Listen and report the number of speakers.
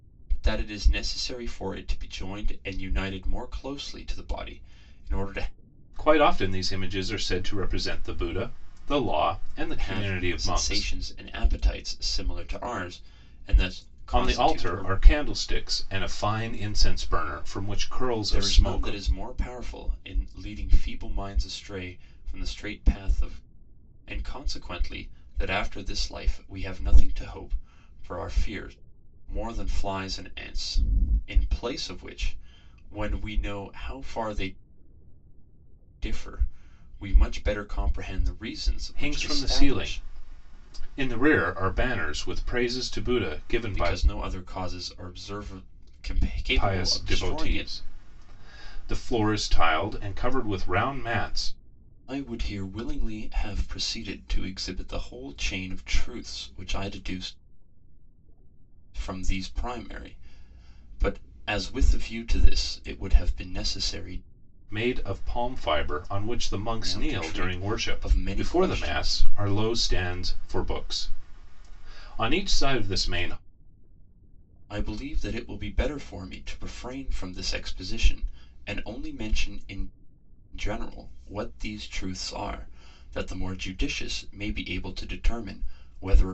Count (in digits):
2